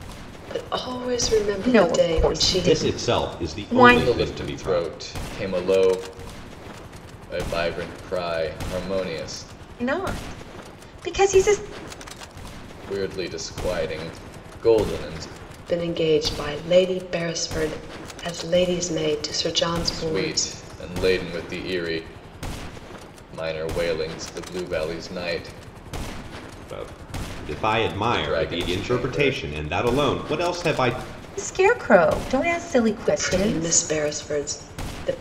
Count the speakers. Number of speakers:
4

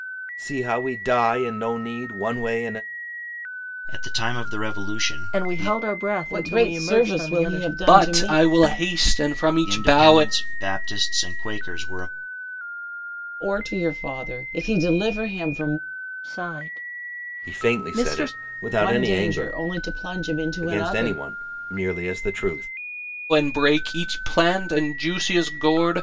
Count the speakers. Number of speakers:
5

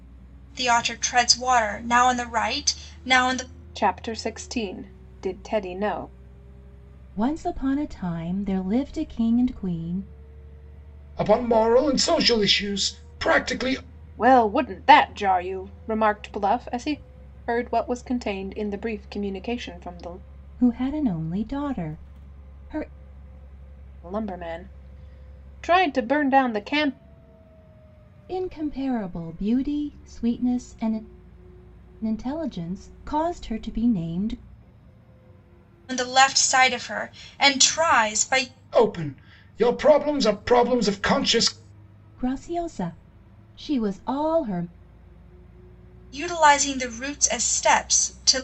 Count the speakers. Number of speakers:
4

